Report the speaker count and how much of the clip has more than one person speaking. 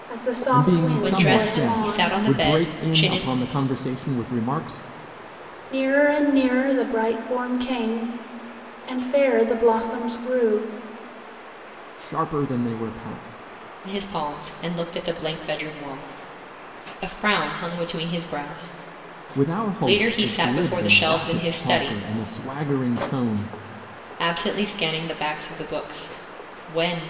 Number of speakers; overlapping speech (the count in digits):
3, about 19%